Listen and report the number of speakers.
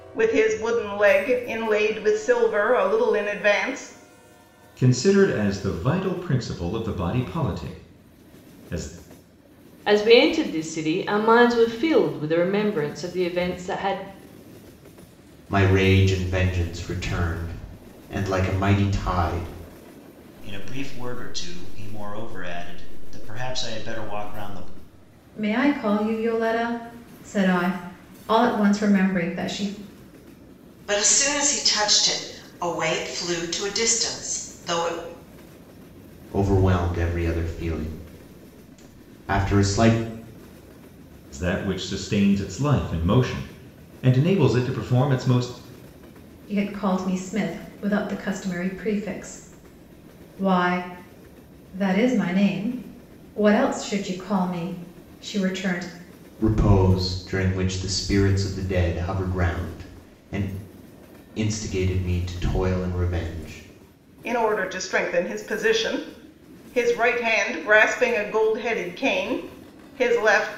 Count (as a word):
seven